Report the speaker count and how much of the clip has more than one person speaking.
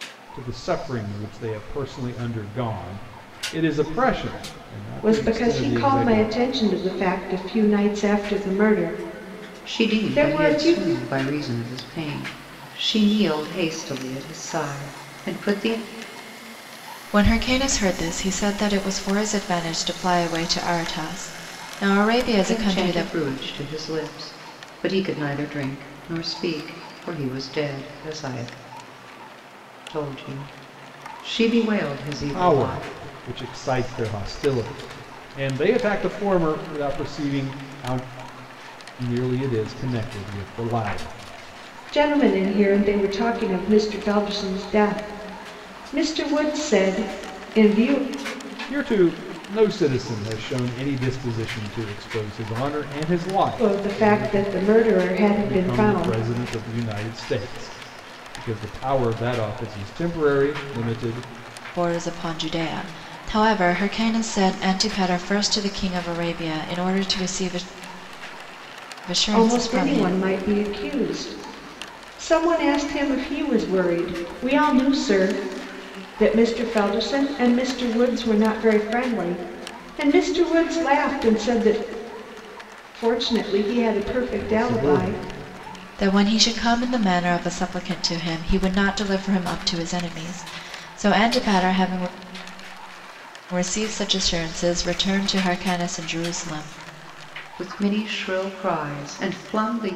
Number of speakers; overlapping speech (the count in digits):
4, about 7%